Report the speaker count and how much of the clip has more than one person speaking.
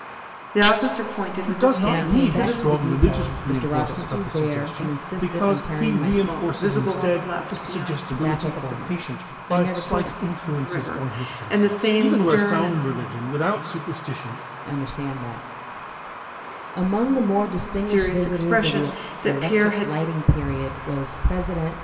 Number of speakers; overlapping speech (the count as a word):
three, about 59%